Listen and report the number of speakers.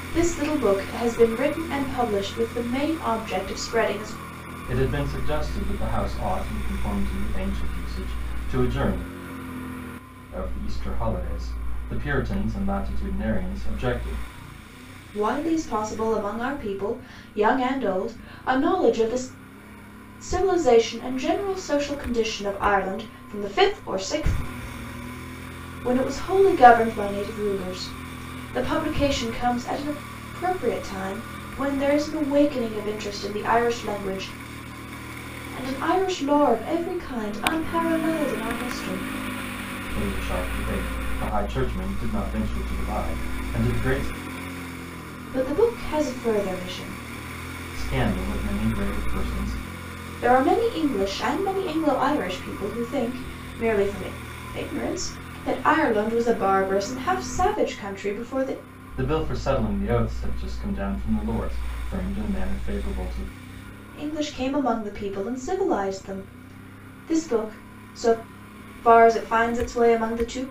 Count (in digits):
2